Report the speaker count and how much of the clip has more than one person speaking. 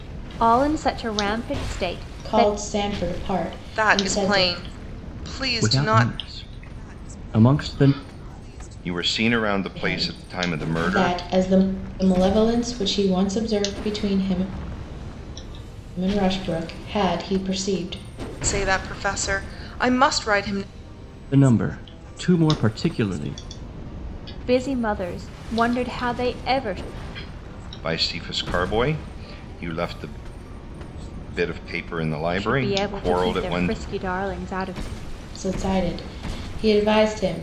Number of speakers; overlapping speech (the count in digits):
5, about 12%